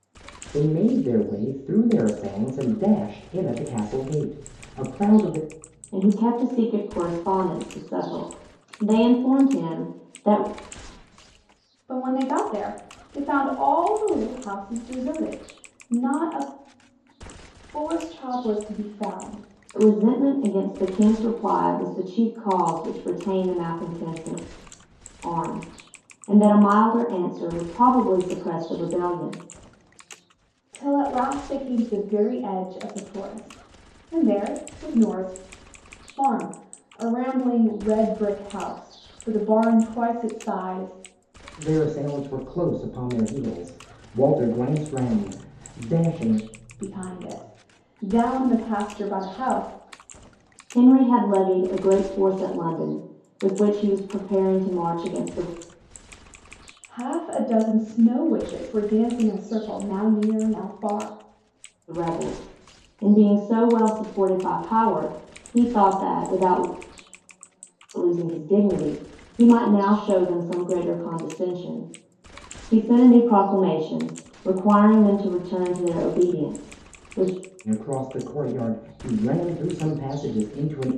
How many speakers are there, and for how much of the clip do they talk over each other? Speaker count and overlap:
3, no overlap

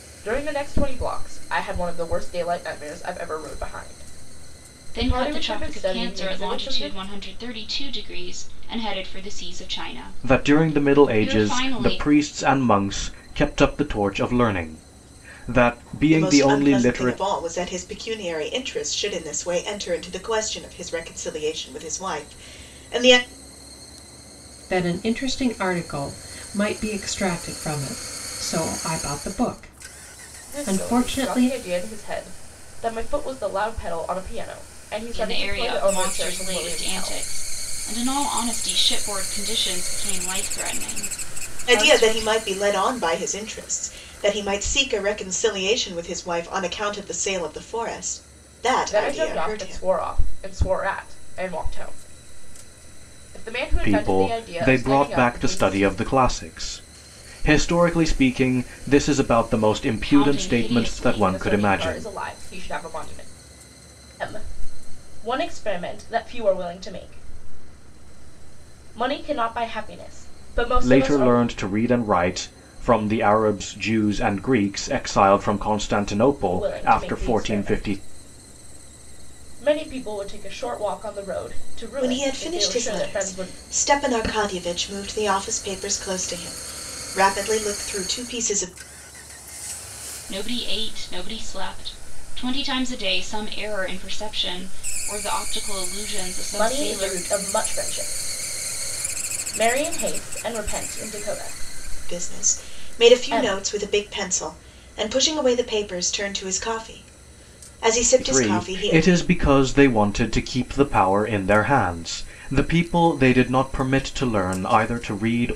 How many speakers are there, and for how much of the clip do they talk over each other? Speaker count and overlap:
5, about 18%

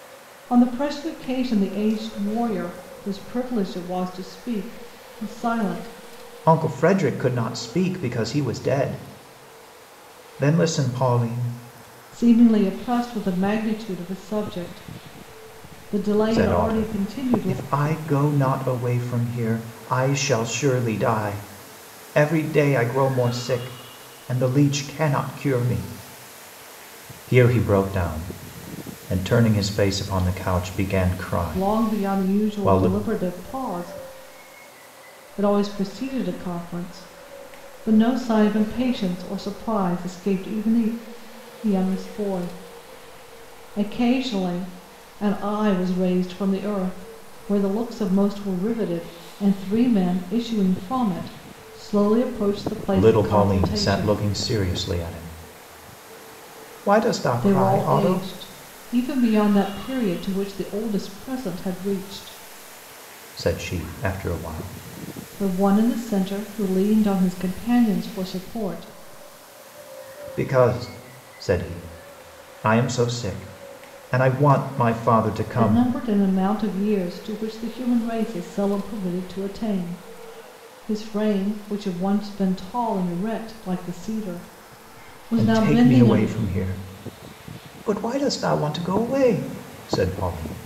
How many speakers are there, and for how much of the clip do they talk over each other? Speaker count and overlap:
2, about 7%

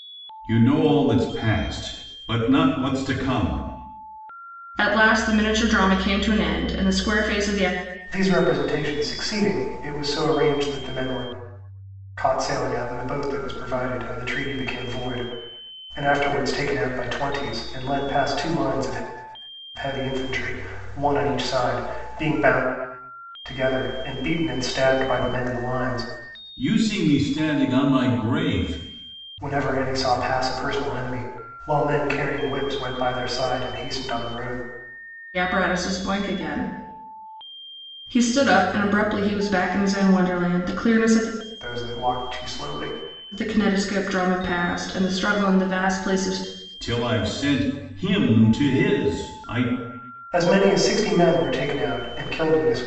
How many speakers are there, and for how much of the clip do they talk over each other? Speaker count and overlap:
3, no overlap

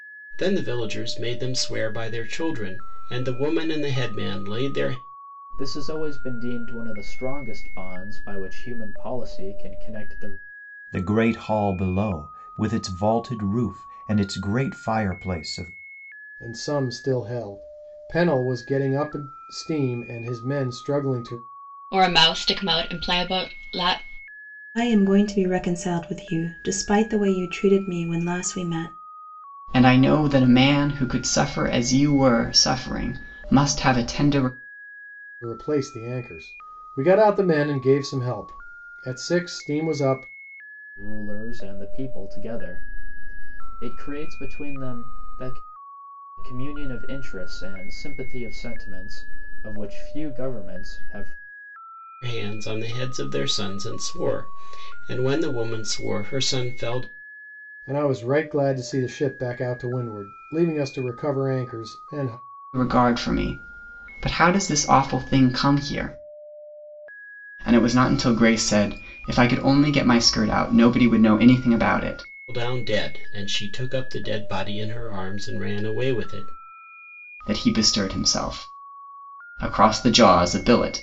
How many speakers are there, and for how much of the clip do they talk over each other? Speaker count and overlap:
7, no overlap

